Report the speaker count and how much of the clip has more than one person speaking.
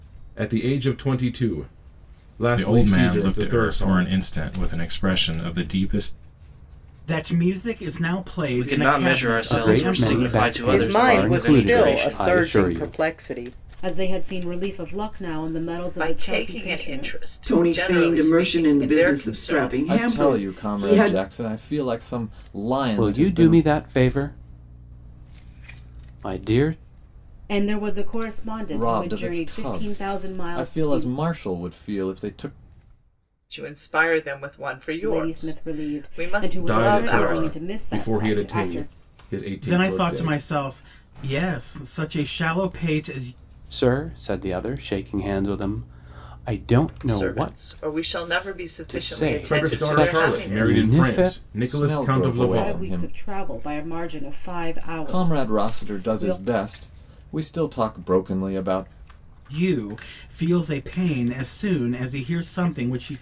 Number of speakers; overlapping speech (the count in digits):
10, about 39%